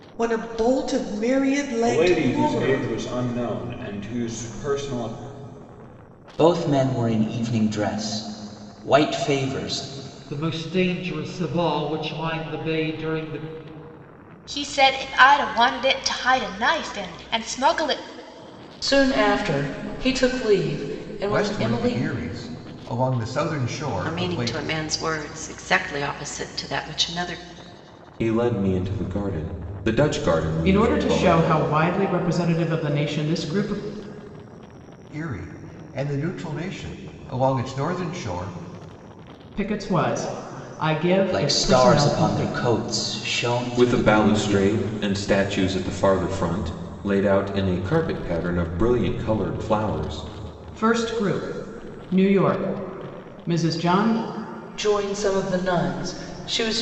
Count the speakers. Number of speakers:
ten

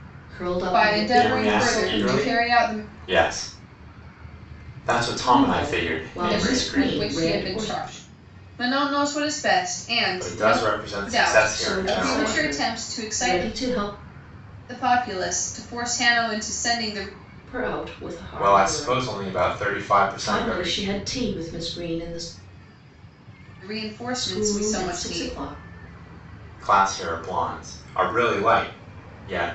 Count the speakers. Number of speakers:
three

